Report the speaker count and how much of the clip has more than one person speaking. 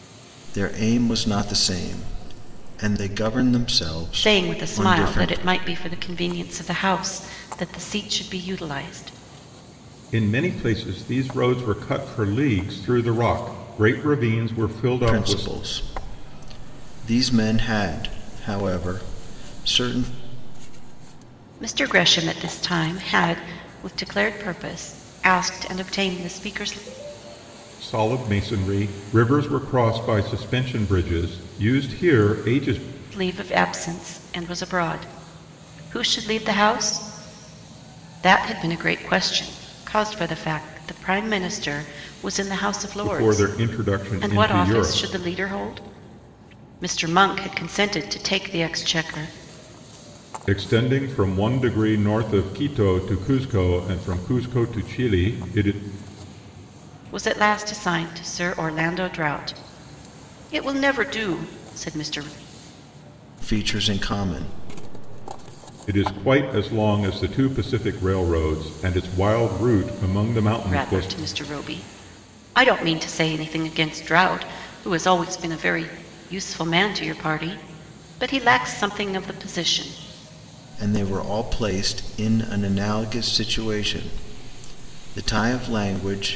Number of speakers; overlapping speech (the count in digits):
3, about 4%